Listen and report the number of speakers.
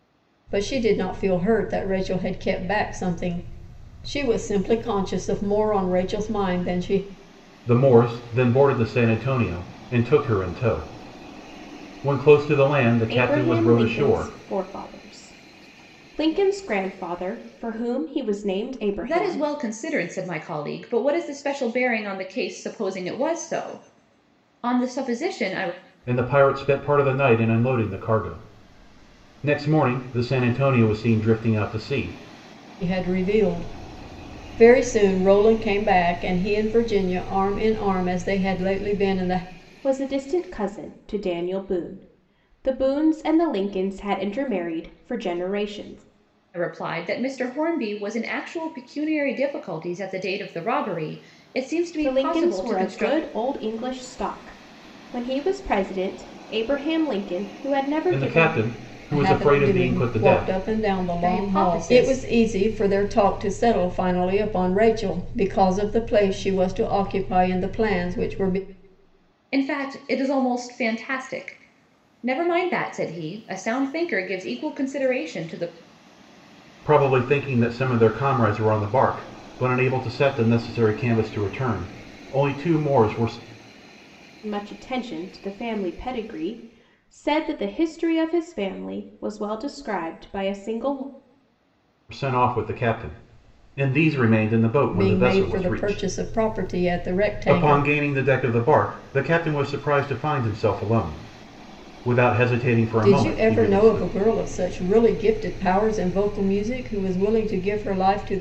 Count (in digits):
4